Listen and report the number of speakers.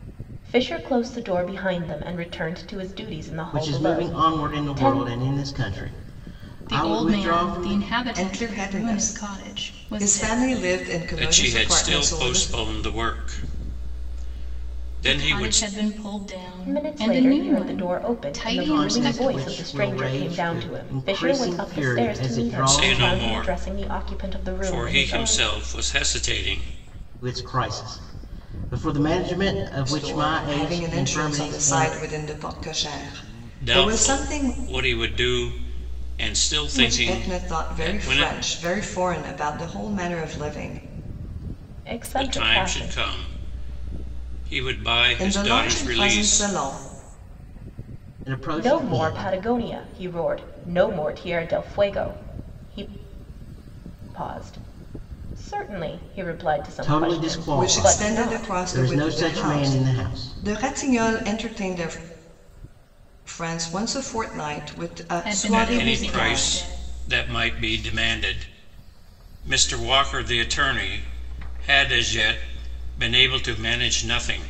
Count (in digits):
5